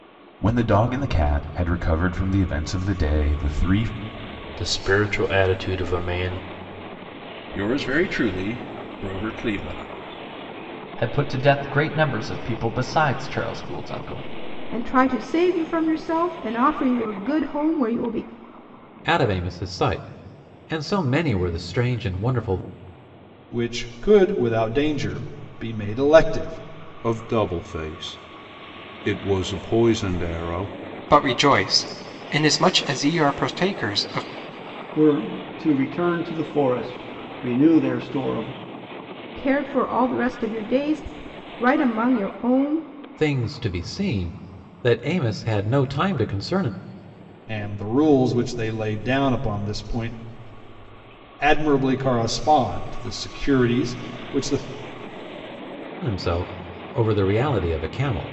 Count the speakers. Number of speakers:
10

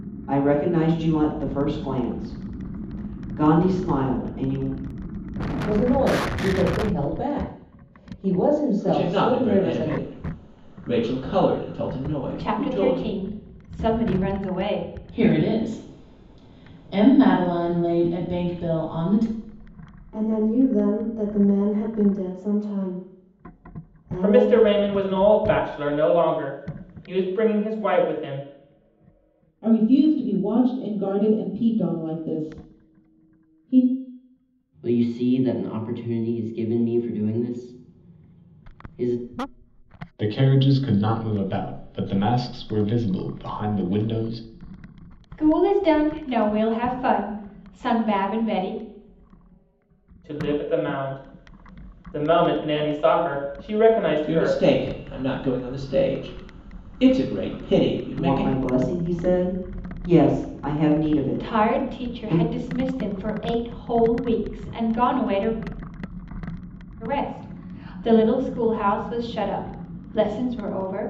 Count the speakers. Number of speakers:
10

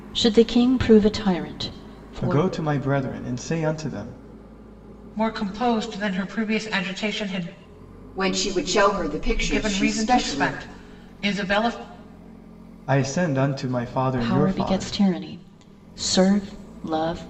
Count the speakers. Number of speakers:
4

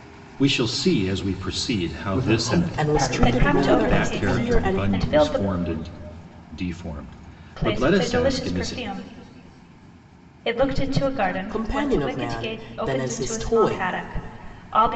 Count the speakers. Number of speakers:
4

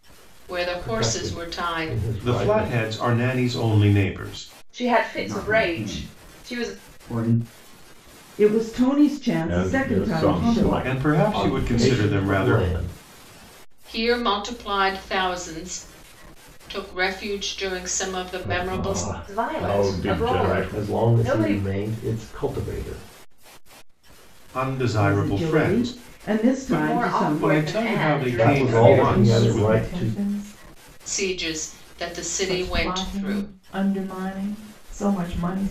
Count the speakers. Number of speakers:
8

